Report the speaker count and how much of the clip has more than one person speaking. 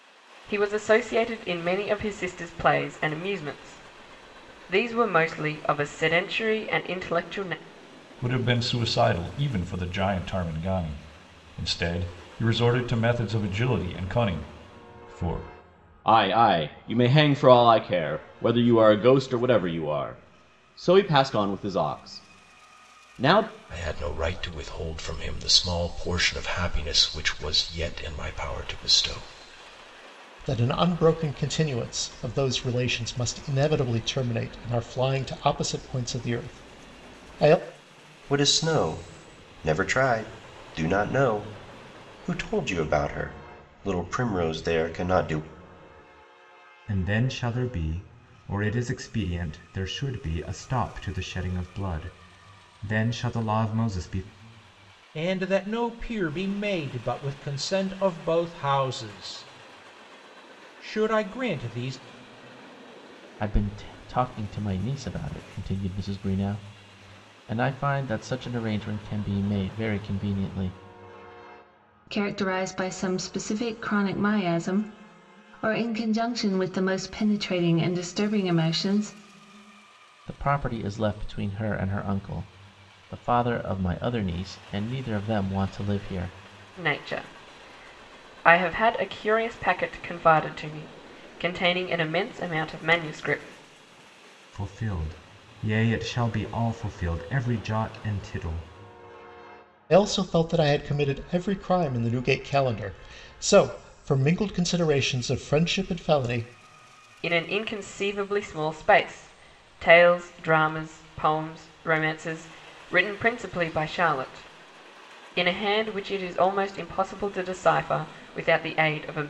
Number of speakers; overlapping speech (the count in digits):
10, no overlap